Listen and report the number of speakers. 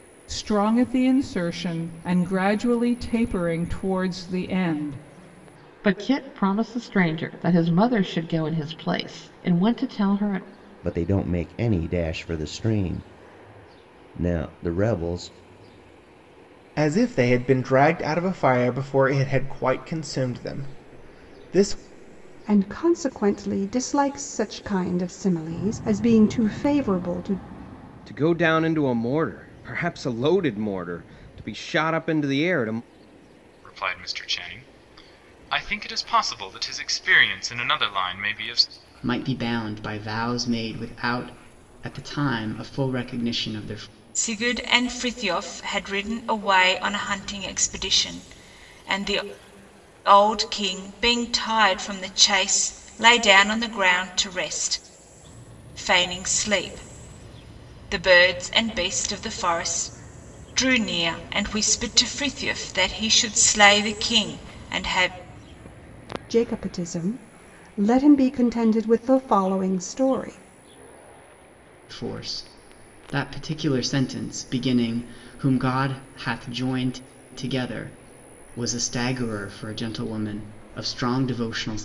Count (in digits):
9